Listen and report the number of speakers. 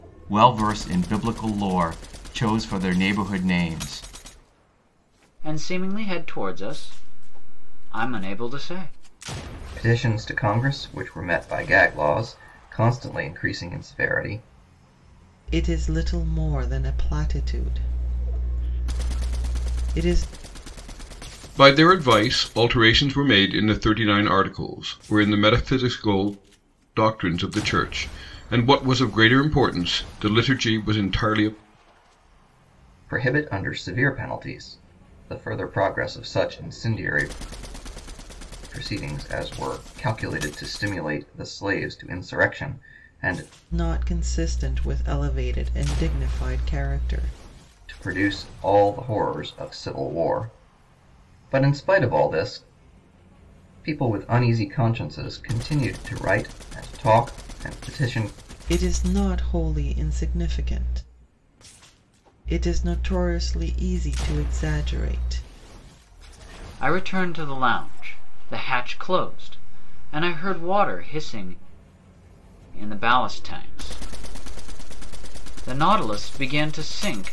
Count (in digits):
5